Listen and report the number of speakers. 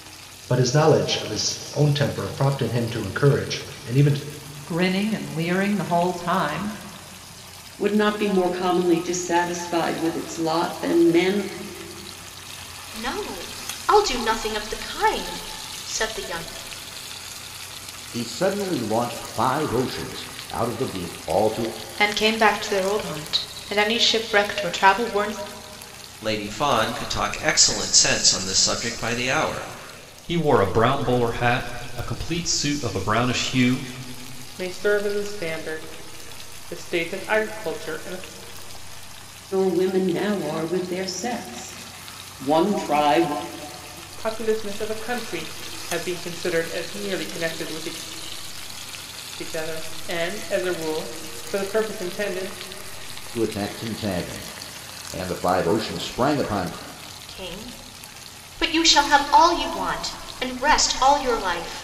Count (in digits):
9